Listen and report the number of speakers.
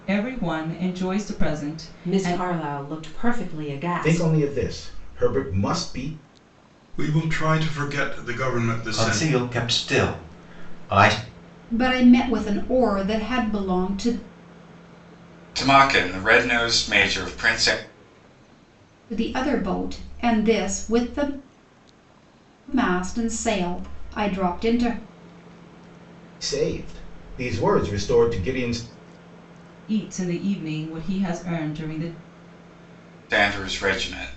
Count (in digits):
7